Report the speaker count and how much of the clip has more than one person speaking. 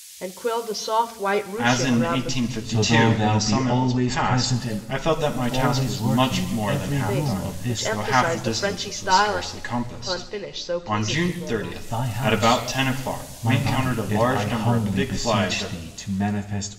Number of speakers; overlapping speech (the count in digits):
3, about 76%